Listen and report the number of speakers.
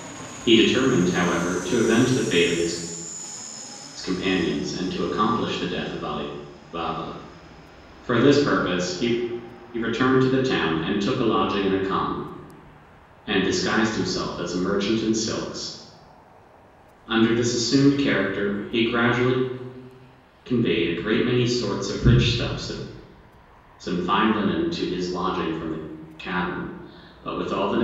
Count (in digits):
1